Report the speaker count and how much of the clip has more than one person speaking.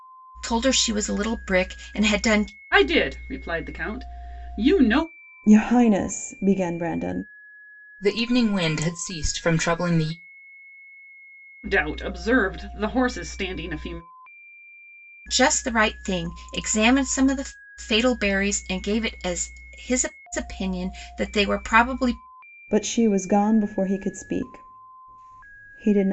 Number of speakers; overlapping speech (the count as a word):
four, no overlap